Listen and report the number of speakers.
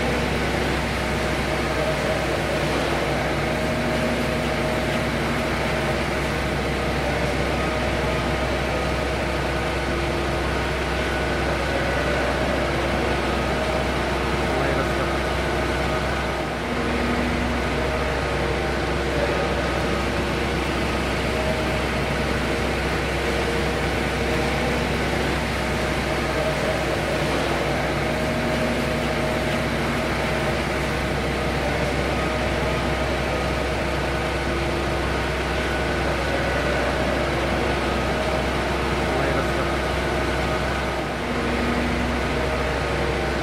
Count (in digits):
0